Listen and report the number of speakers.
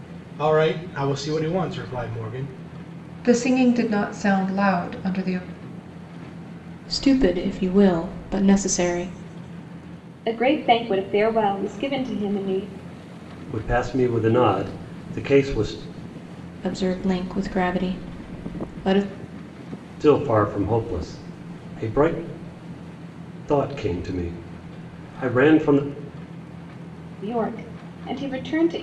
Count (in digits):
5